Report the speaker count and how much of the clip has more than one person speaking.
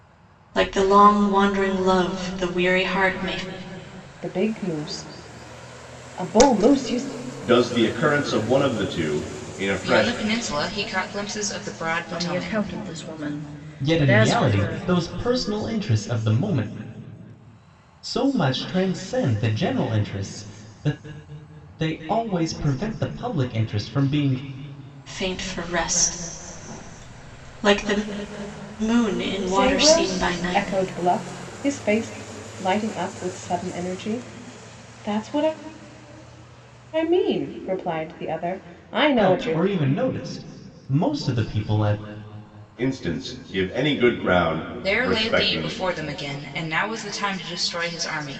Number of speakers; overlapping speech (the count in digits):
6, about 10%